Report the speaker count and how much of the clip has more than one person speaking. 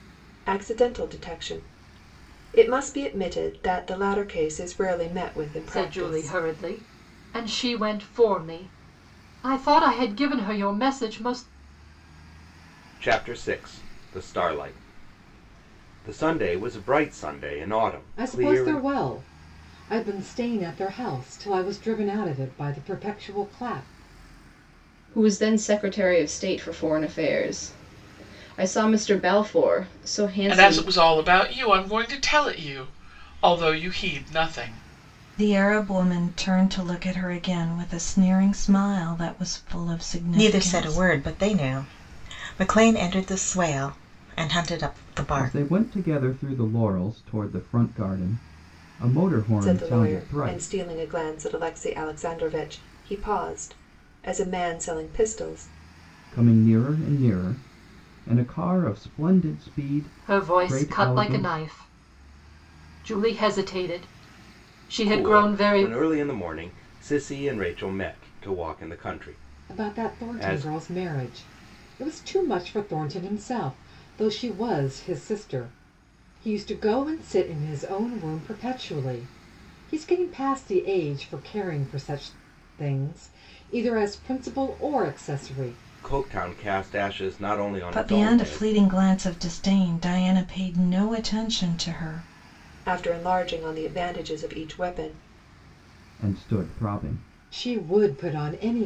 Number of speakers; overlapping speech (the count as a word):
nine, about 9%